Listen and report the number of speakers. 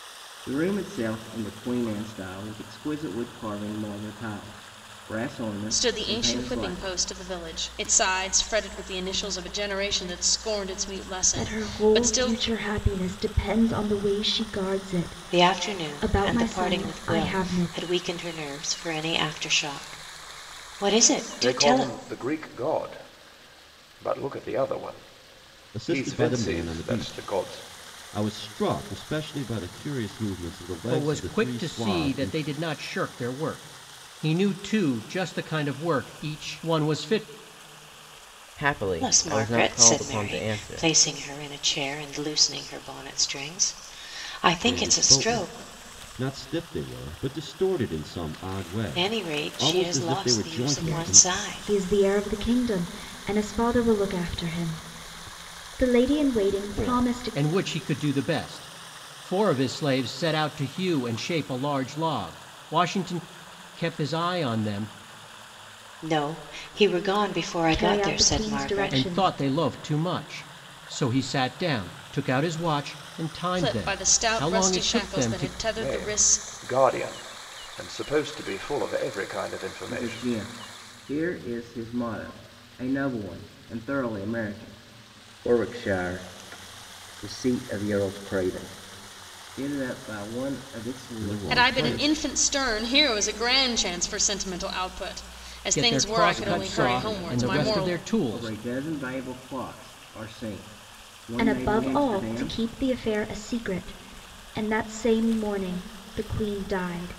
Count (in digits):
8